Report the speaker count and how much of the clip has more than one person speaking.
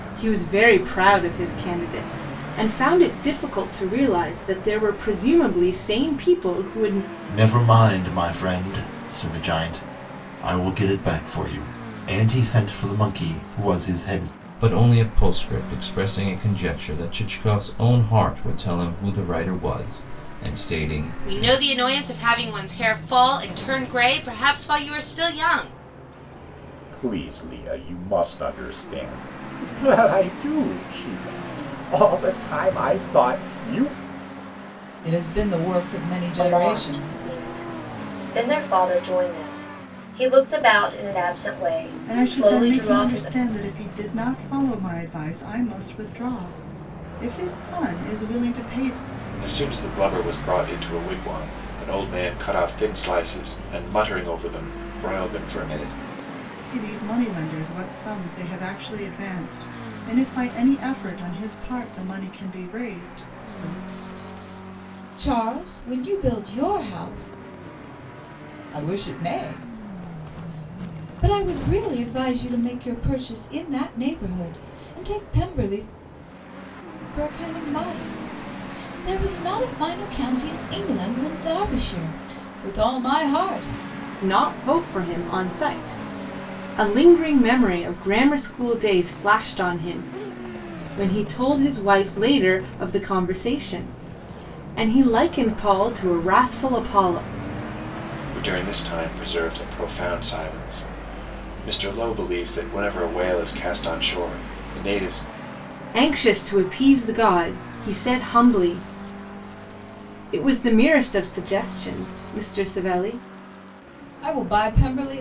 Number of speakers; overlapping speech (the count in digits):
9, about 2%